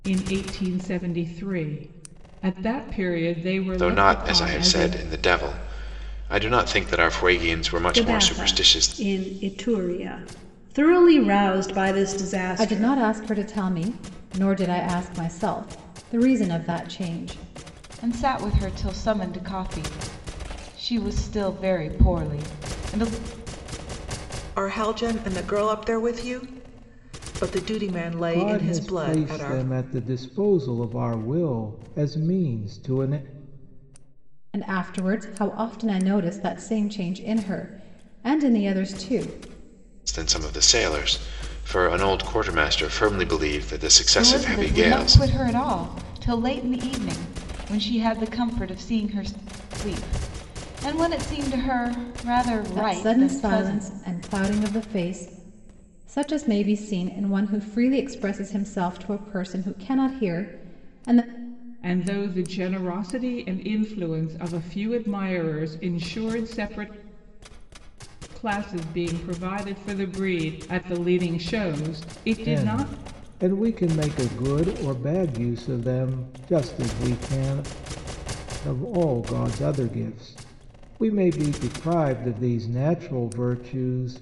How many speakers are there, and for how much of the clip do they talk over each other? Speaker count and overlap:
seven, about 8%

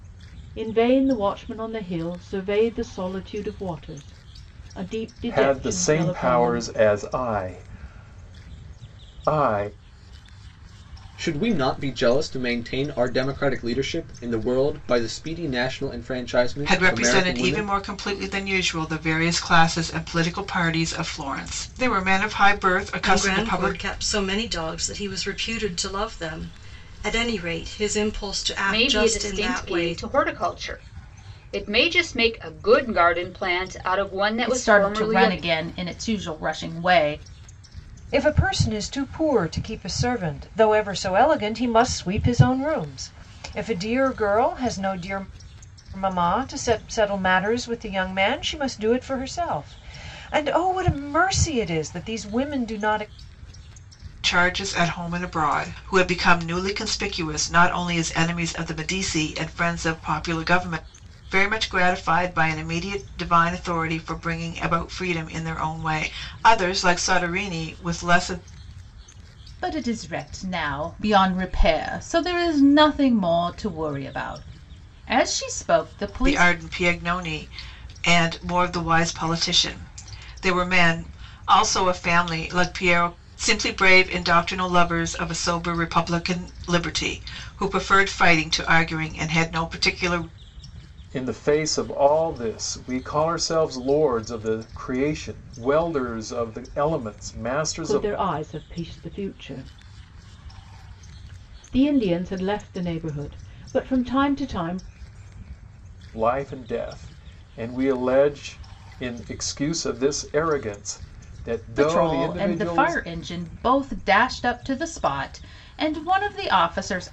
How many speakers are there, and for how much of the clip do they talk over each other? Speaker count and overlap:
eight, about 7%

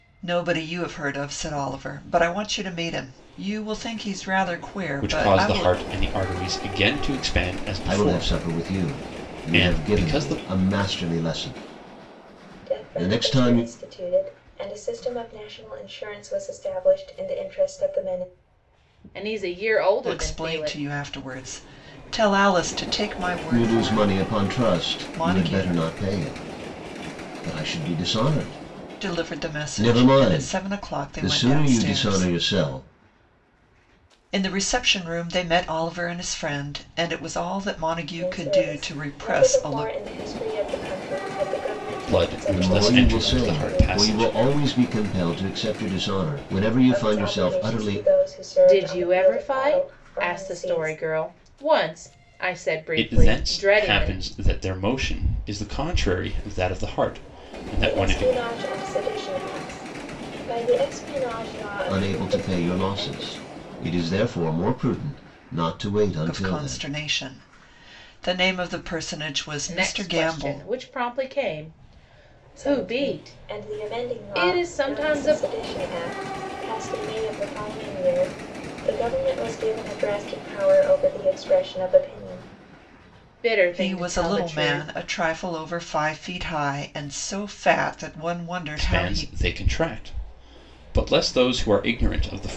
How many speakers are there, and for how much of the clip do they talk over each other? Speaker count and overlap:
five, about 30%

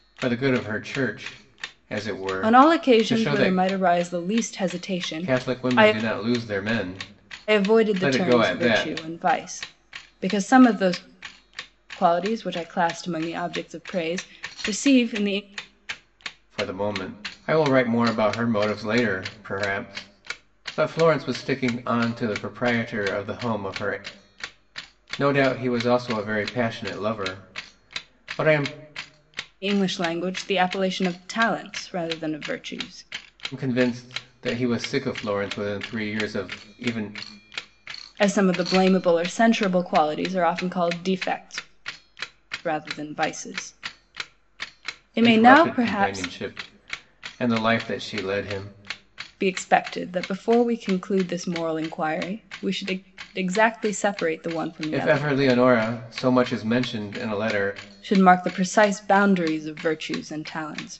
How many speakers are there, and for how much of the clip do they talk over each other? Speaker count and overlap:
two, about 8%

